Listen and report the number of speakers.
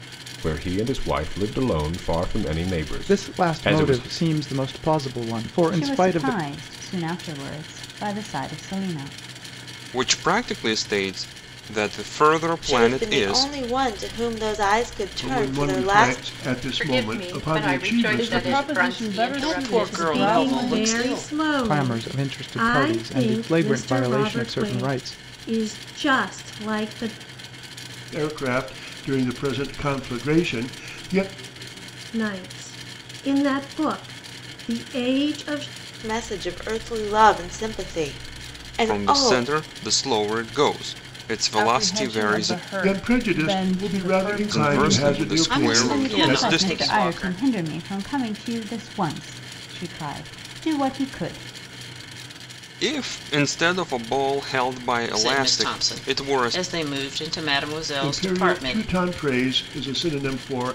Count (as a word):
ten